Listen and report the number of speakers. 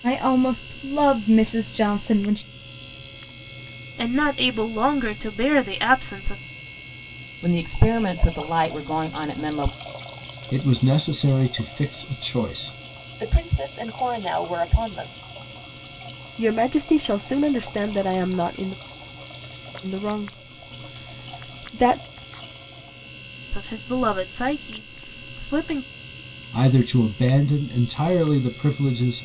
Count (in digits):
6